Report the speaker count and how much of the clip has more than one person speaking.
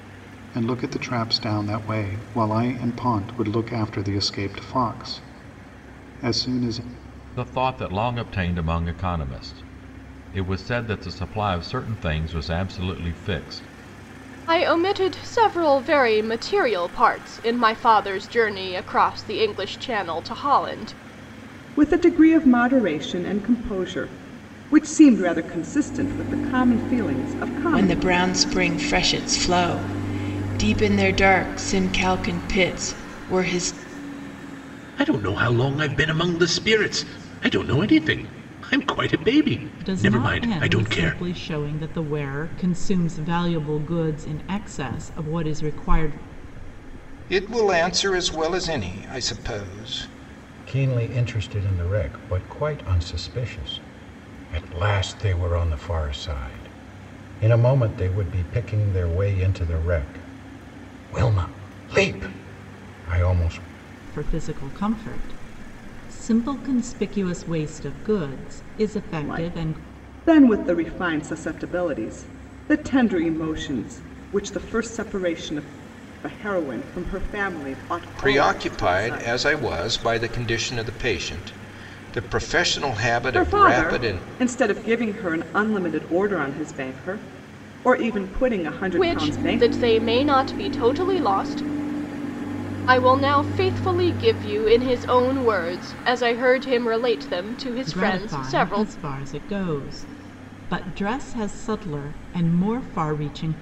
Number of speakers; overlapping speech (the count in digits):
9, about 6%